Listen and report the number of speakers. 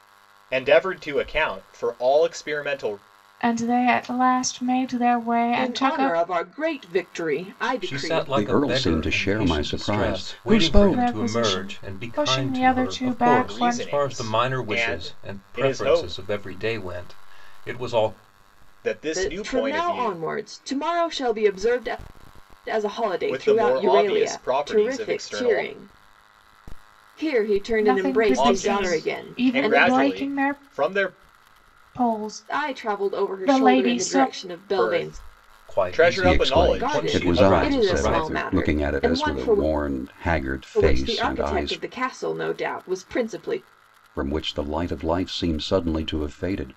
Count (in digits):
5